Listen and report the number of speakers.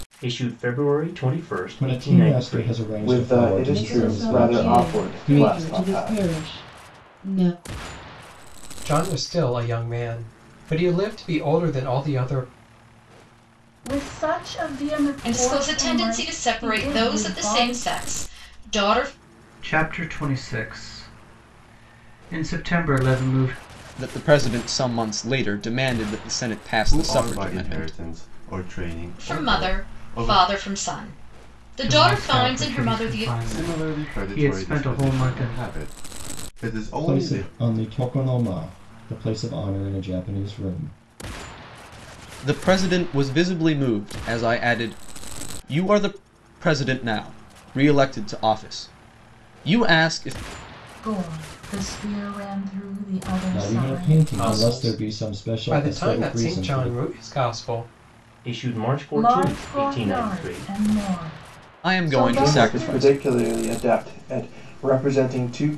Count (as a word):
ten